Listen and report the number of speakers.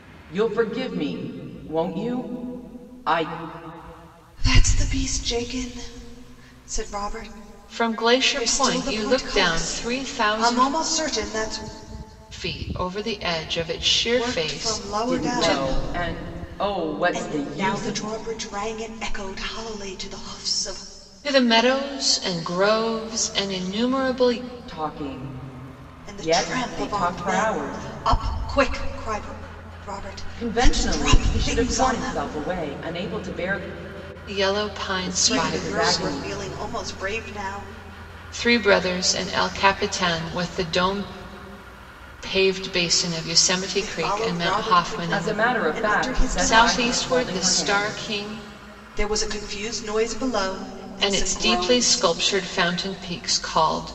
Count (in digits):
3